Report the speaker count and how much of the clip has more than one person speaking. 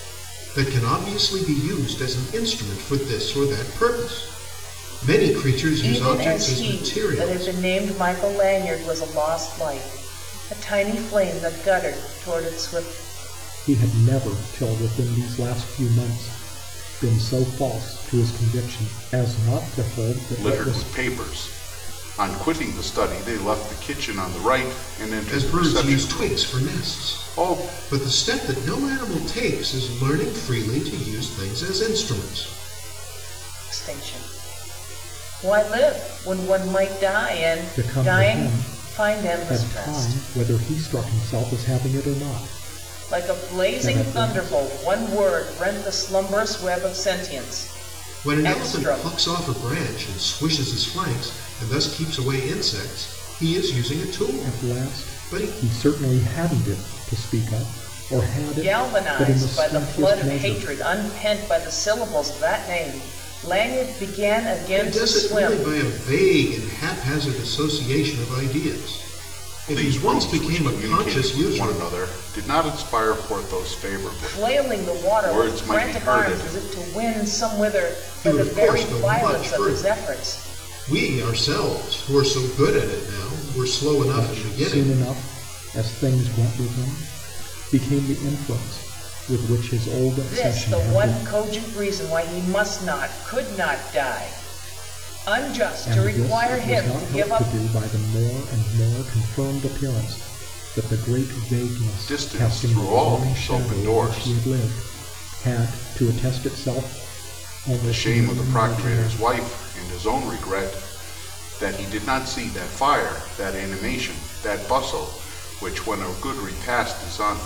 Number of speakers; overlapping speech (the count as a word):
four, about 24%